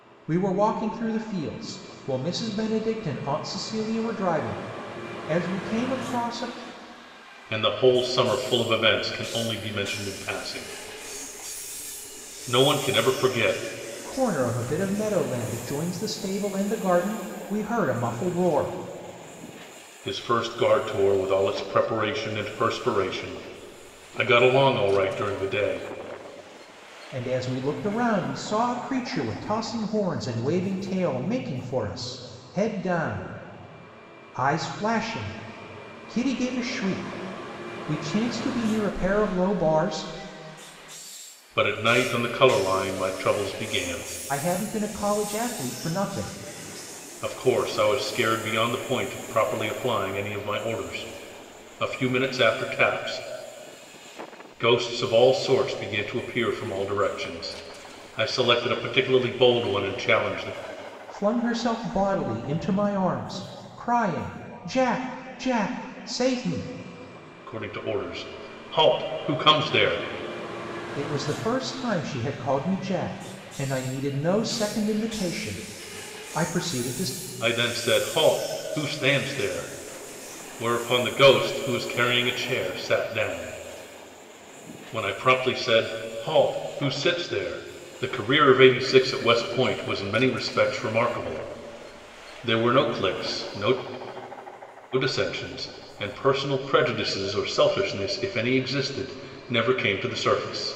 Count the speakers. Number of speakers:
2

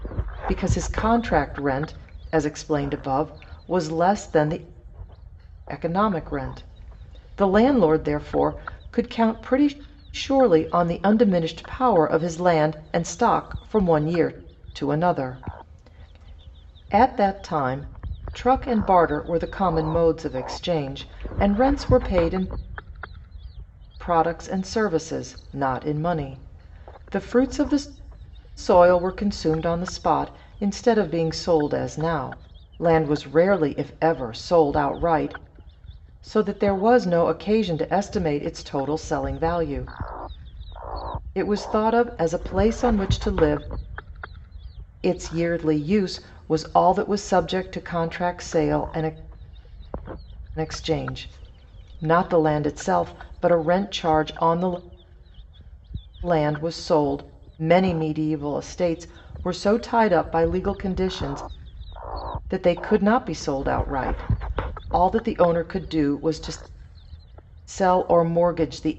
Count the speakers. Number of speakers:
1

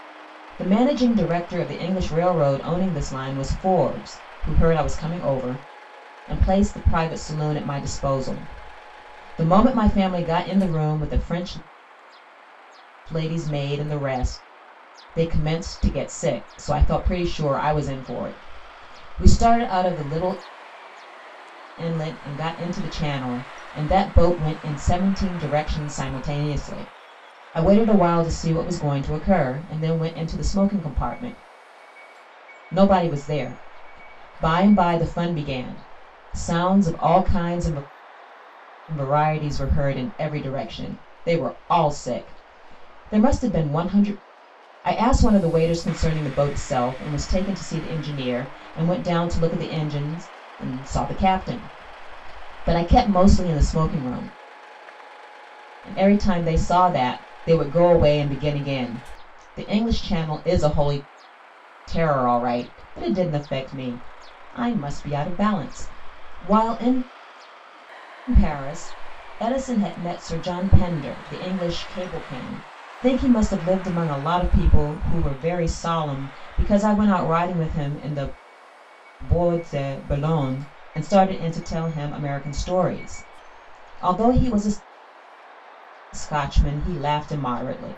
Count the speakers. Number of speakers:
1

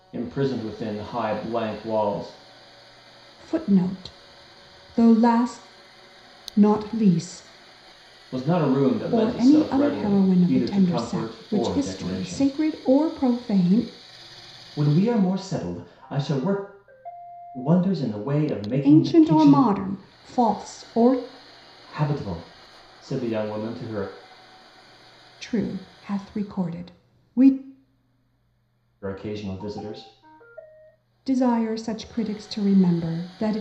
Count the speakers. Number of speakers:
2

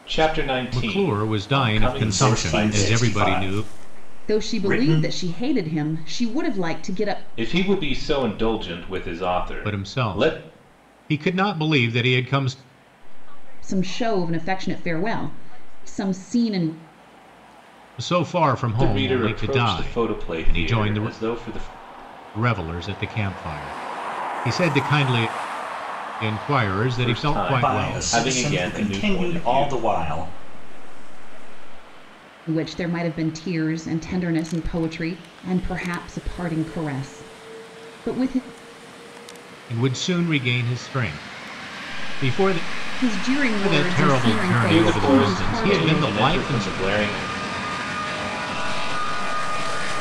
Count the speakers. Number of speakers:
5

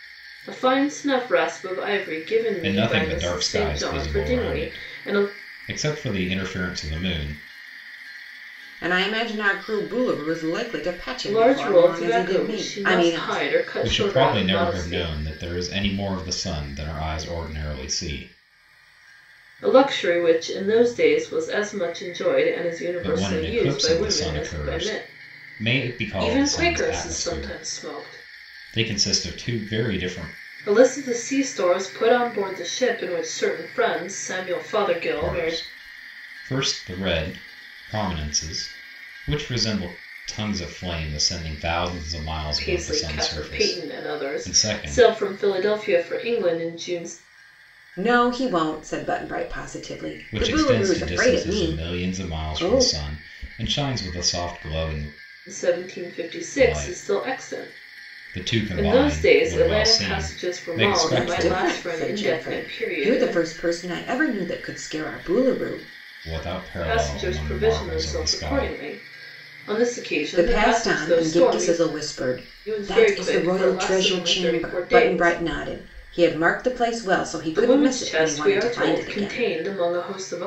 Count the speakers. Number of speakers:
3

